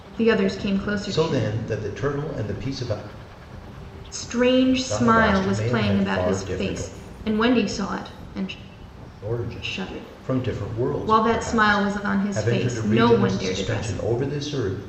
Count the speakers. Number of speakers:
two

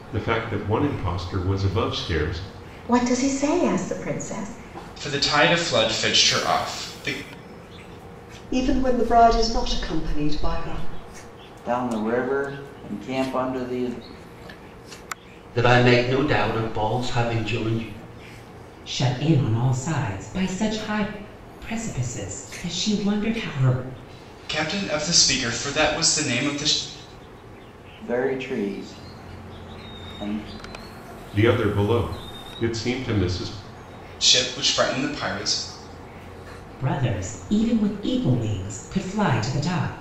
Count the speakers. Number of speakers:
seven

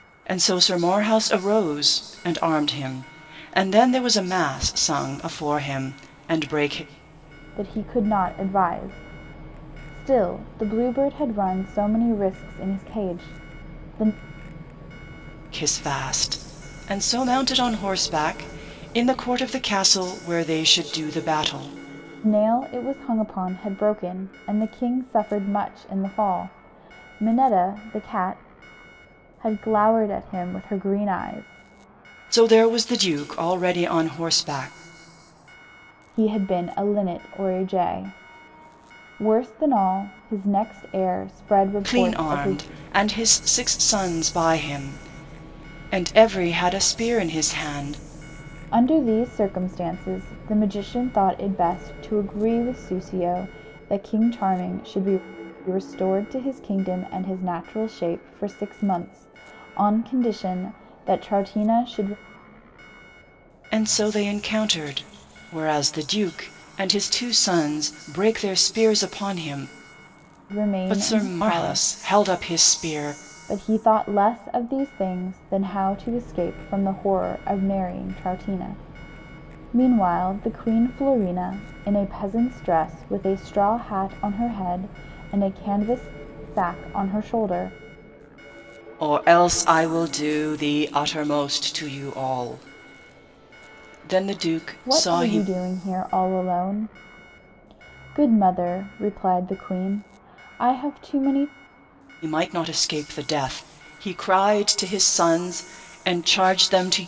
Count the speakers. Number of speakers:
two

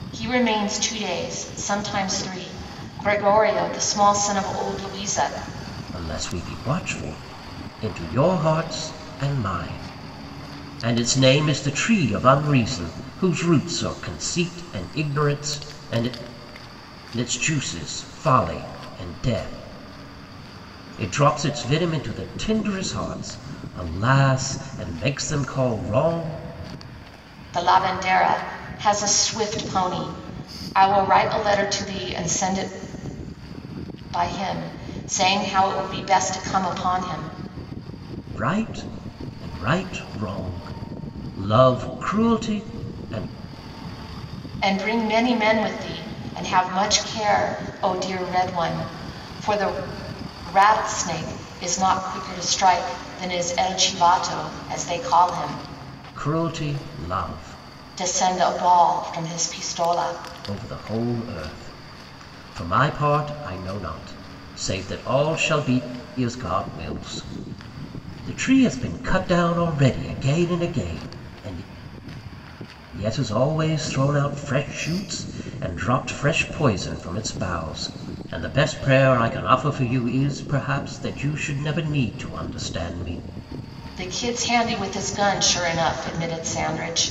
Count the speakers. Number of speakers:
two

